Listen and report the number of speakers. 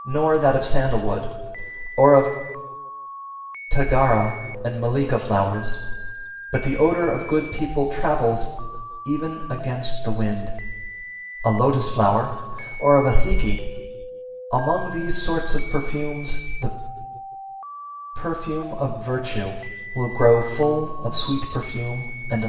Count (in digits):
1